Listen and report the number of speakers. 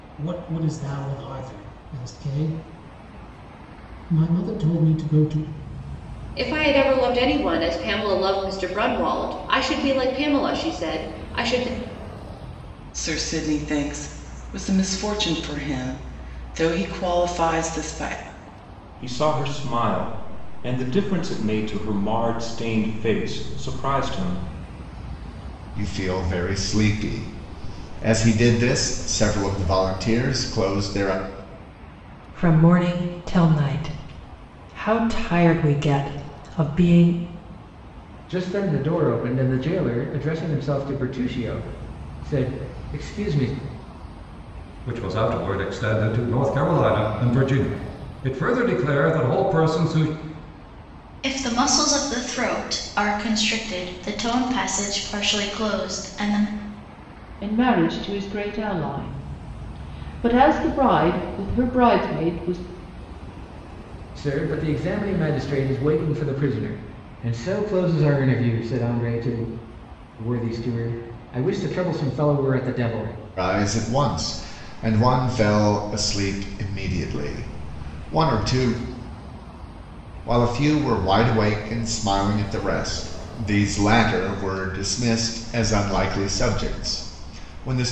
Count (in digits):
10